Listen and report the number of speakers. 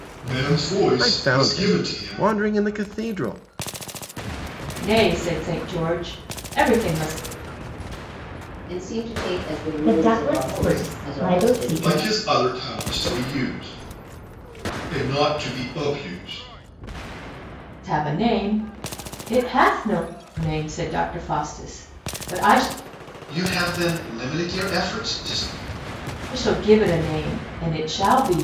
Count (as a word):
five